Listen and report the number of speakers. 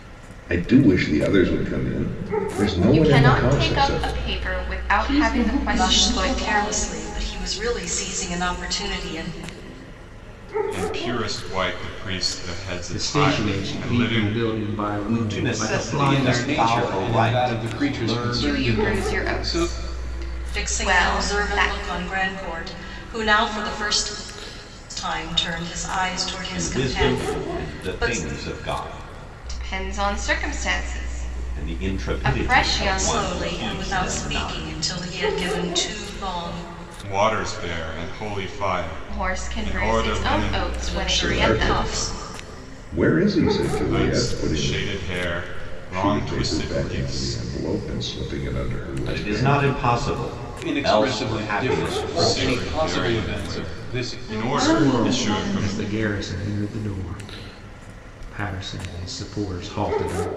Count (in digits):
8